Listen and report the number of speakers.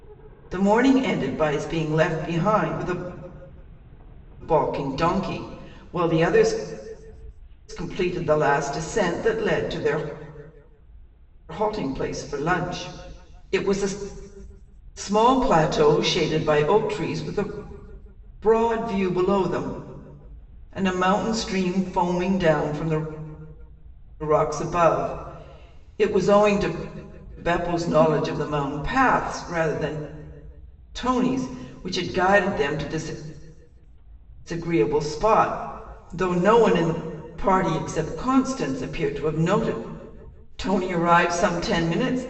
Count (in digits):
1